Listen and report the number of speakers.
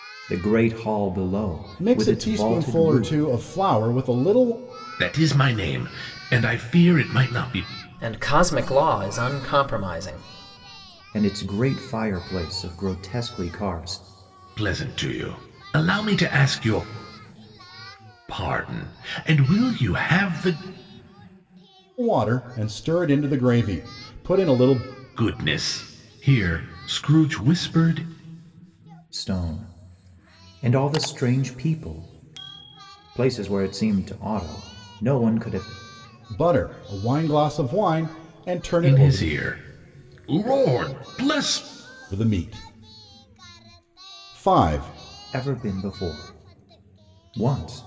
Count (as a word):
four